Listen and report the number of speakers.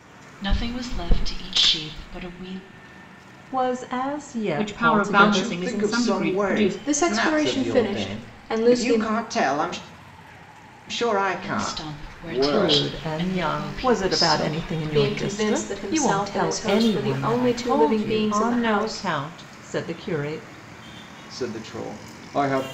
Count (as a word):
five